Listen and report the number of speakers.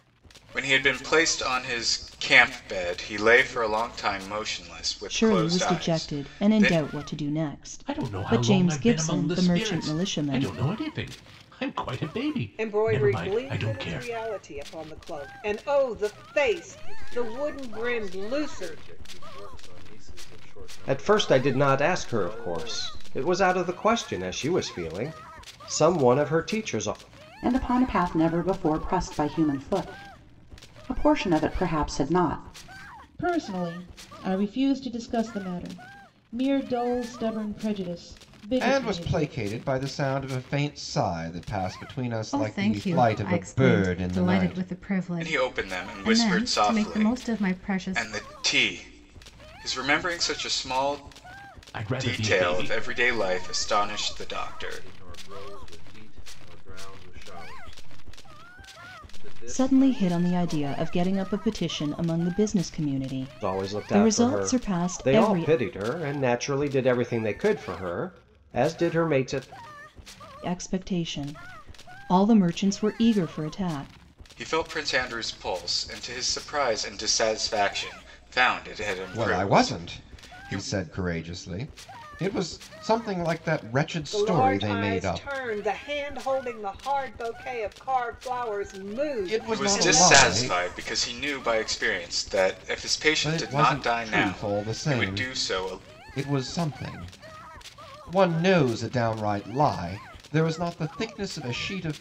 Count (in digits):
10